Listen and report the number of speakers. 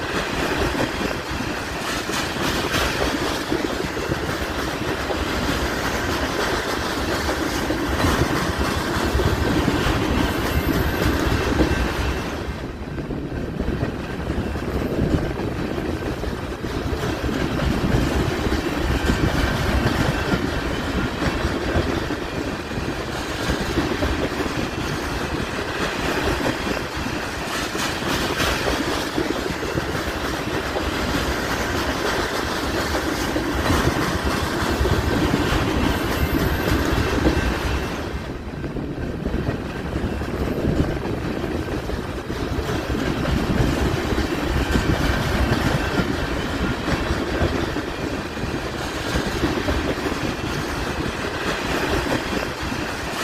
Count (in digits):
0